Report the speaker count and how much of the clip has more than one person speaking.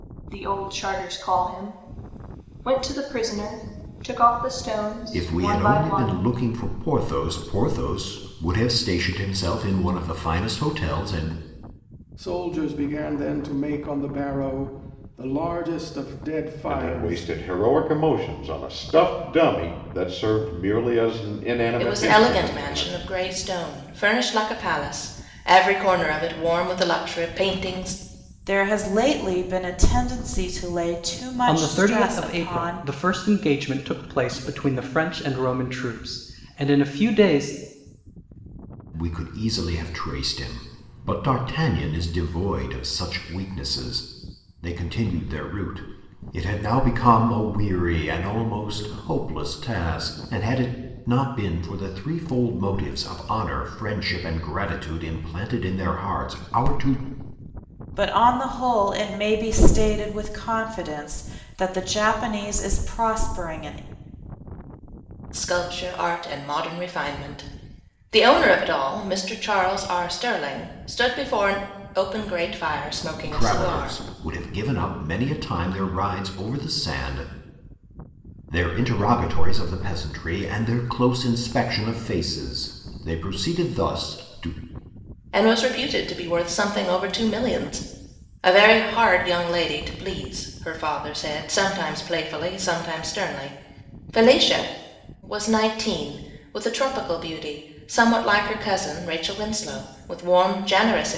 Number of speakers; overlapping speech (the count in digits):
7, about 5%